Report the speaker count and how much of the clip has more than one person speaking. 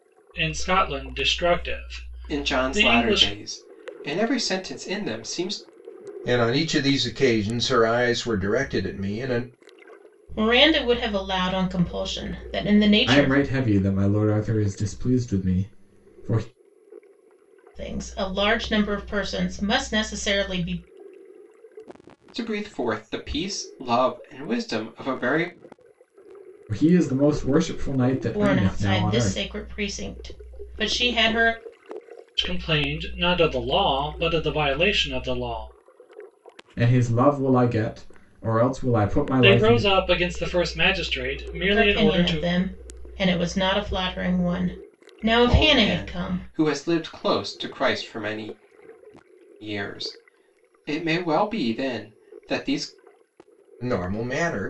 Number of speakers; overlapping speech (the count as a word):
five, about 9%